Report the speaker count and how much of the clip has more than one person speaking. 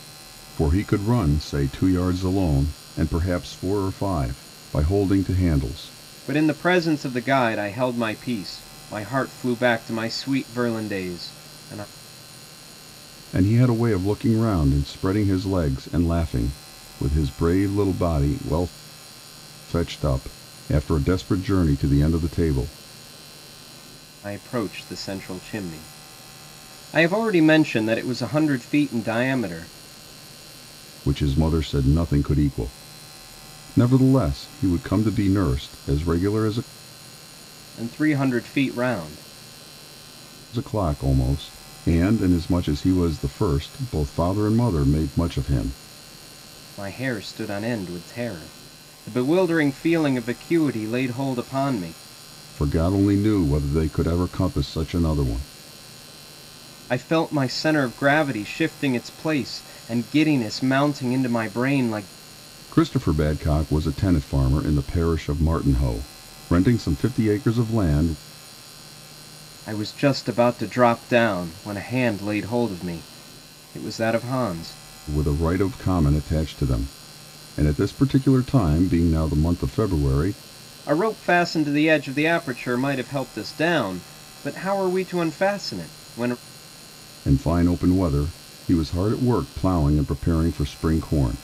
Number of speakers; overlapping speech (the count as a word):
two, no overlap